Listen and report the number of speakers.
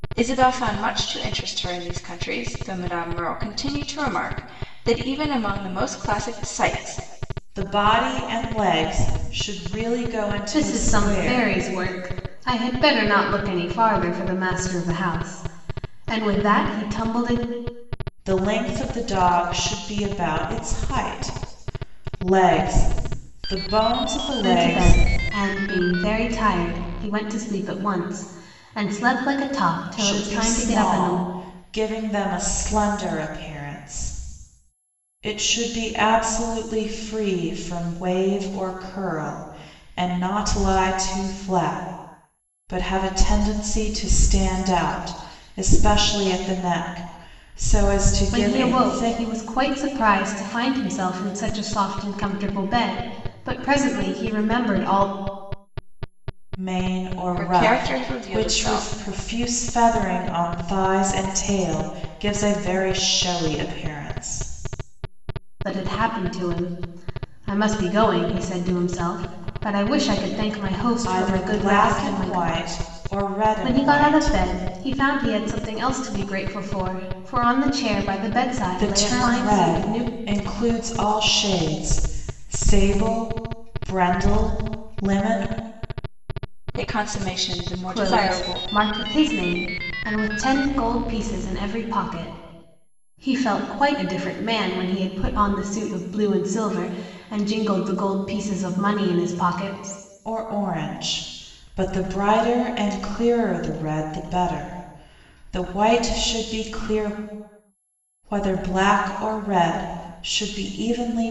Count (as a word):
three